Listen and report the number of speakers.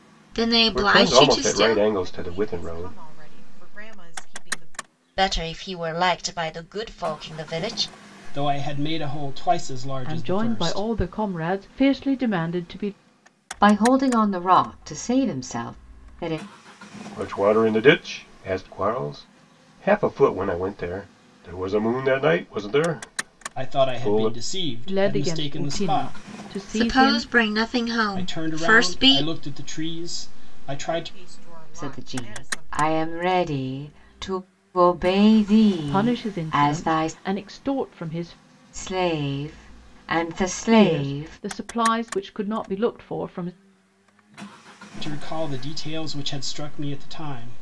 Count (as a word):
seven